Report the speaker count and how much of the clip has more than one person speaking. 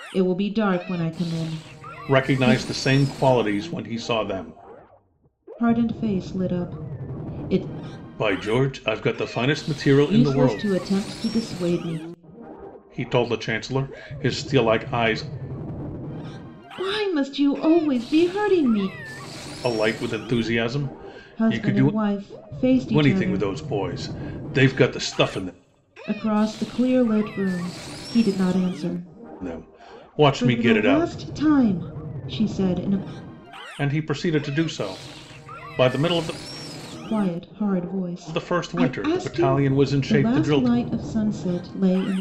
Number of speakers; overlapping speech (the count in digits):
2, about 15%